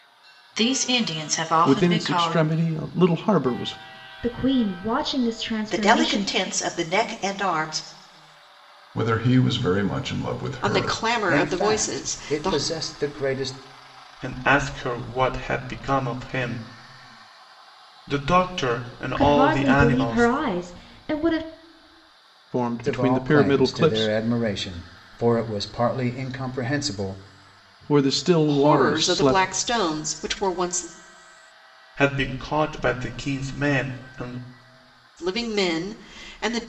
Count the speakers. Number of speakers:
8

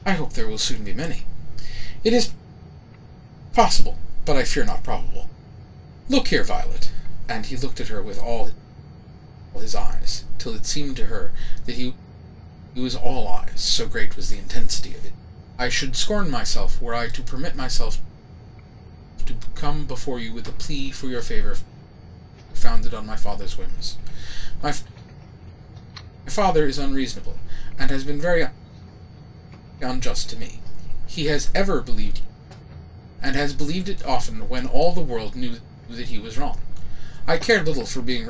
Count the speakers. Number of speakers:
1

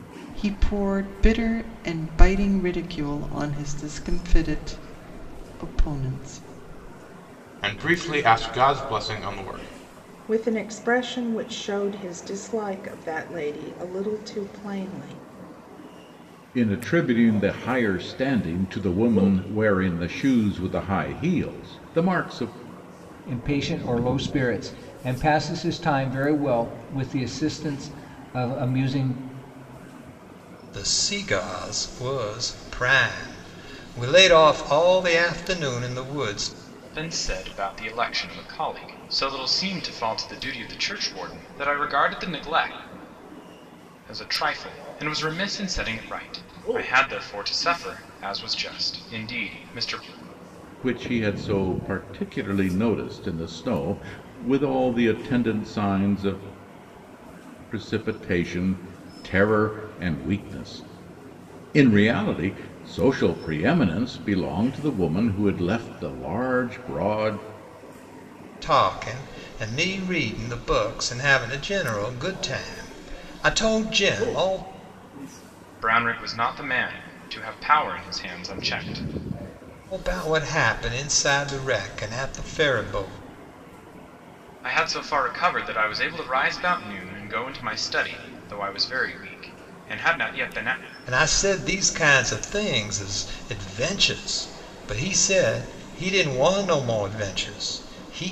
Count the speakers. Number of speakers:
7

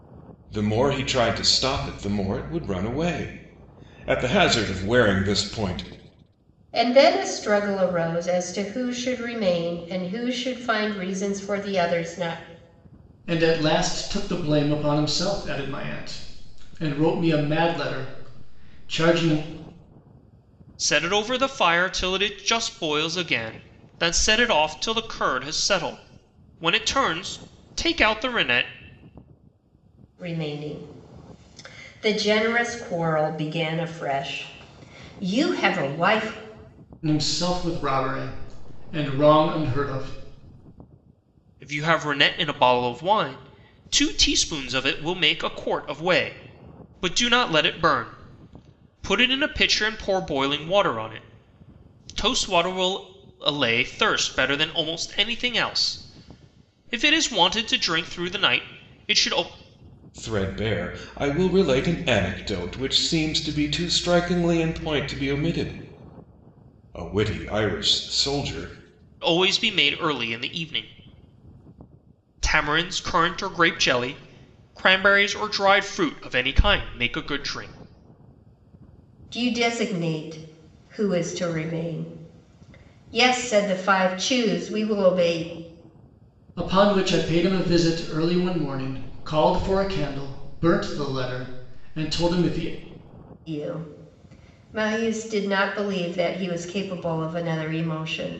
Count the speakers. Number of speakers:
4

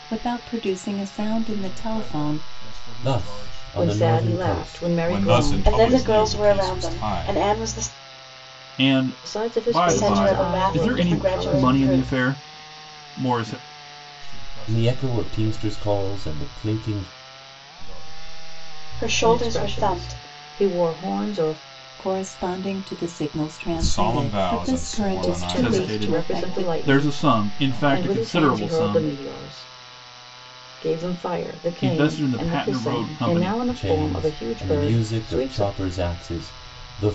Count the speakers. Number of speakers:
7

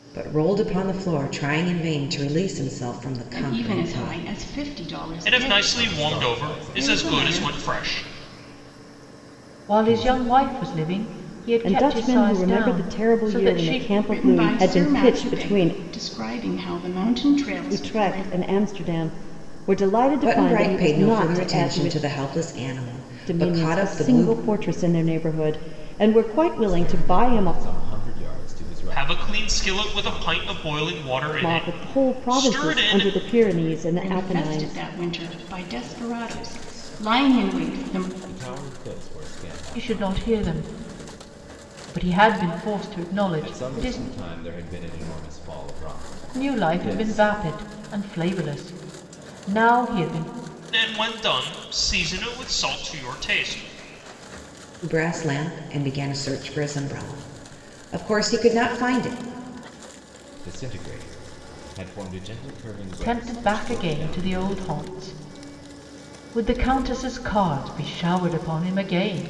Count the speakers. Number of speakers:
6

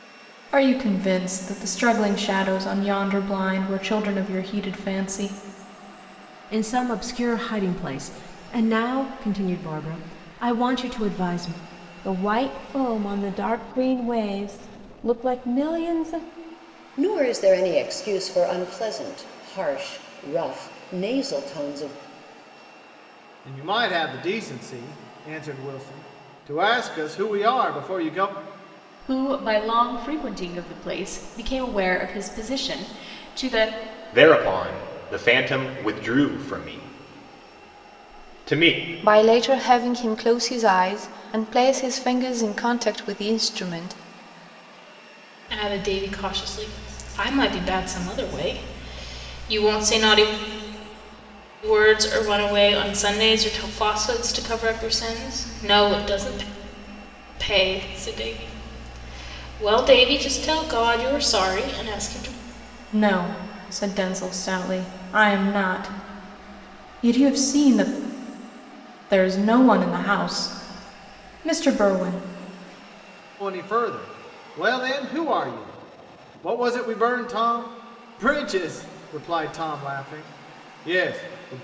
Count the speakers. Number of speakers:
9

